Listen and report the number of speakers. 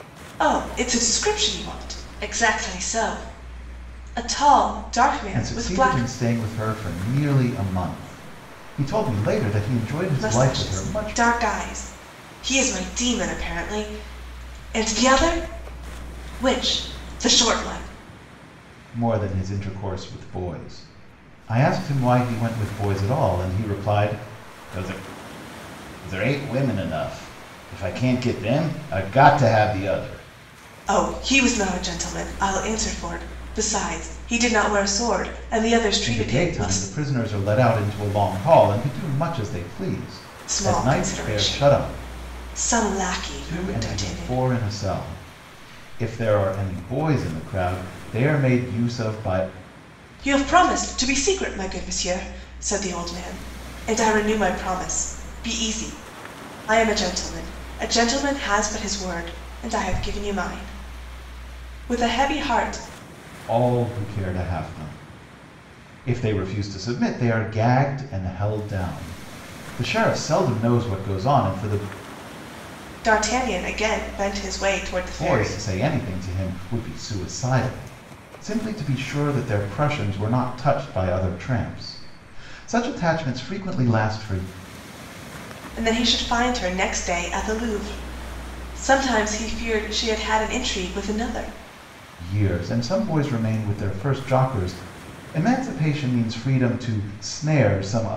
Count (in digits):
2